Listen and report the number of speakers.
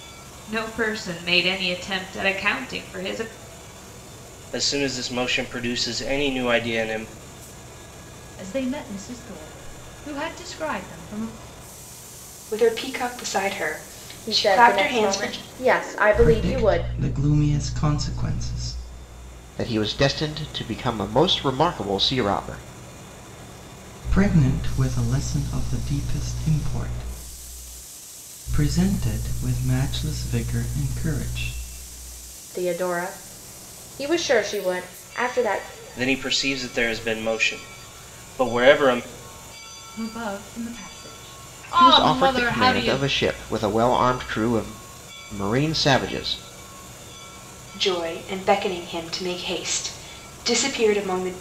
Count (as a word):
seven